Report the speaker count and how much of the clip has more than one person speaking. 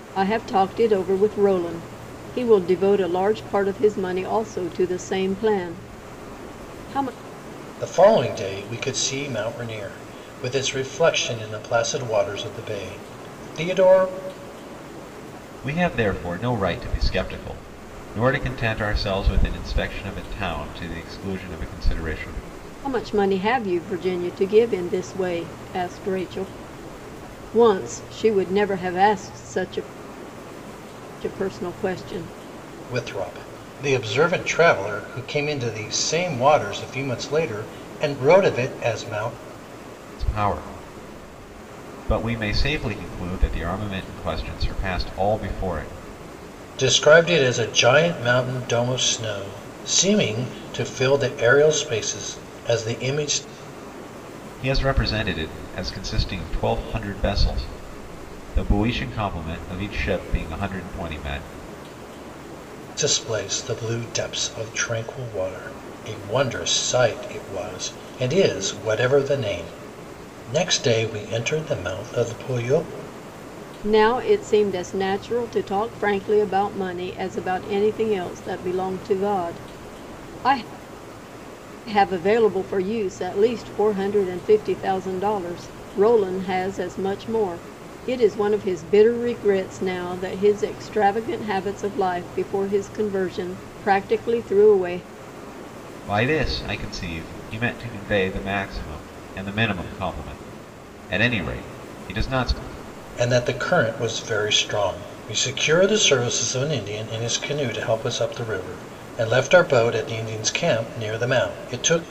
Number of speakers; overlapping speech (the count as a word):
three, no overlap